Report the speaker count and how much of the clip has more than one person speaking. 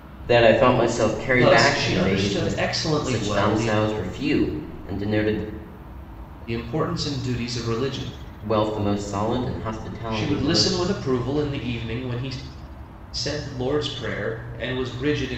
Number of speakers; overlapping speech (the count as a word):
two, about 18%